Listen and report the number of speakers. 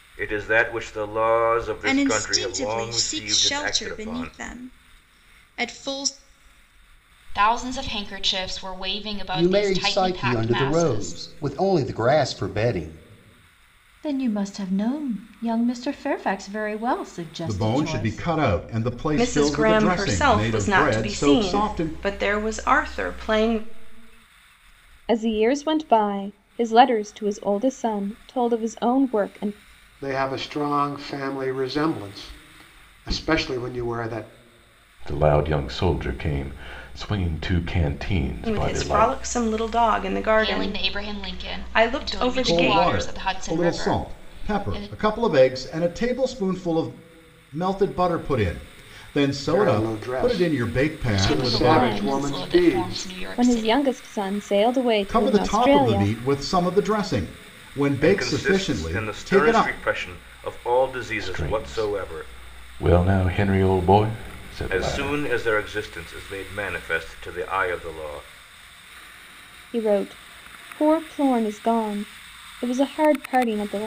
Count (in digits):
10